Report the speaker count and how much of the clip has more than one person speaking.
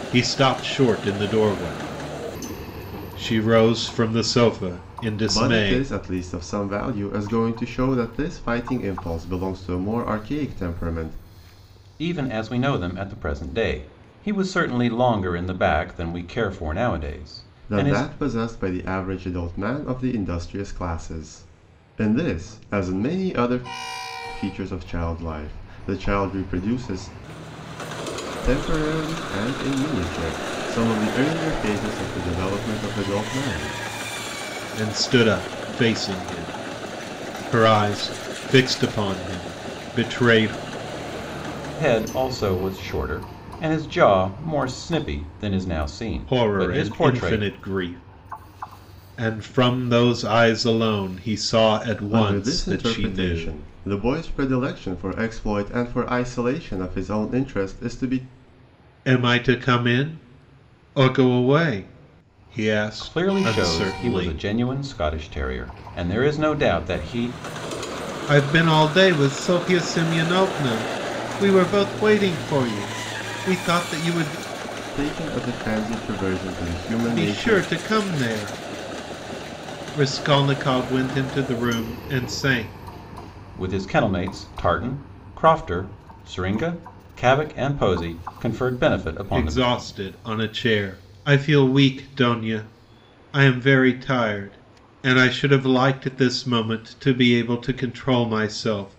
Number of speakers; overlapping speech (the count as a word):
three, about 6%